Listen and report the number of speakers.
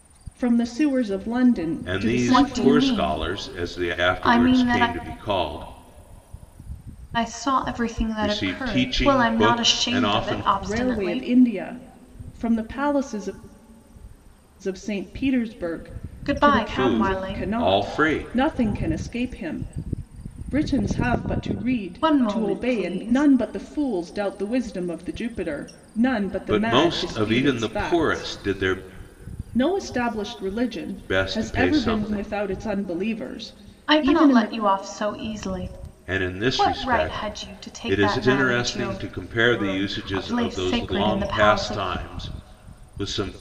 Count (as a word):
three